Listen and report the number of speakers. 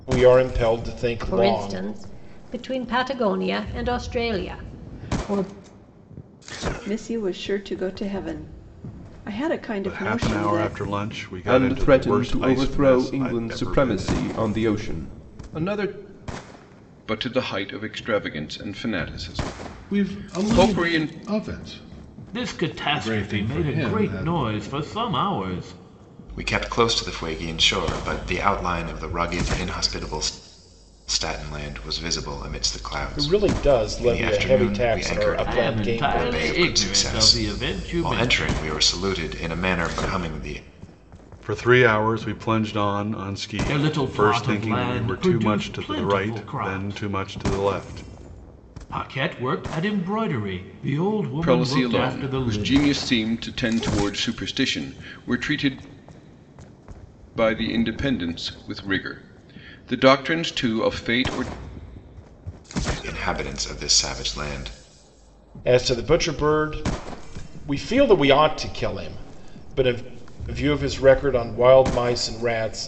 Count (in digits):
9